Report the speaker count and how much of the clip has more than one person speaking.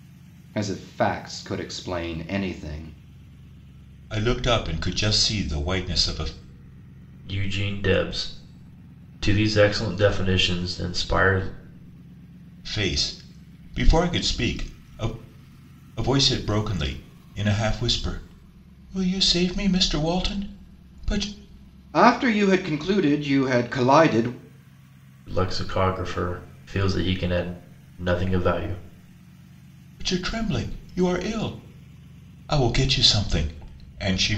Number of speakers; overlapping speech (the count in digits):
3, no overlap